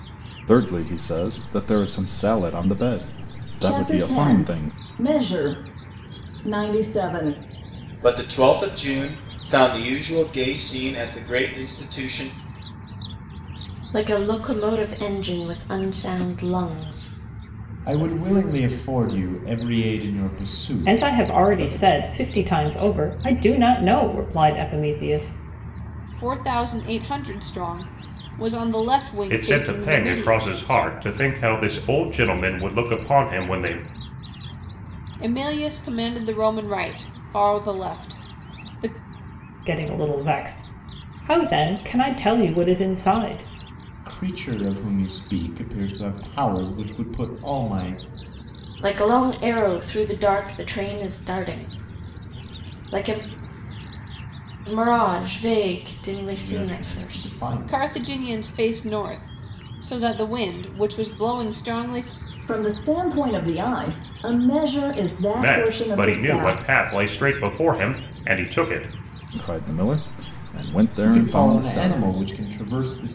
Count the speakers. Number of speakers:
8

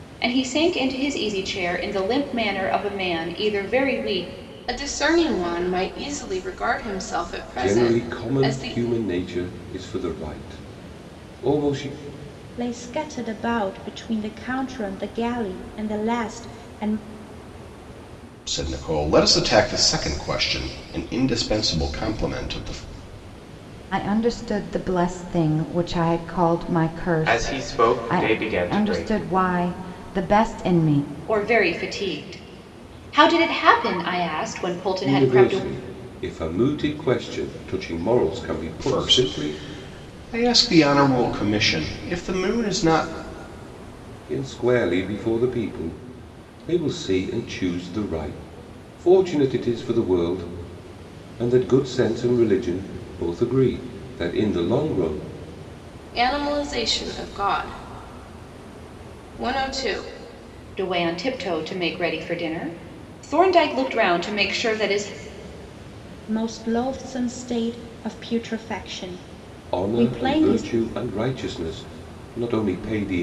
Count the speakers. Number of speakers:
7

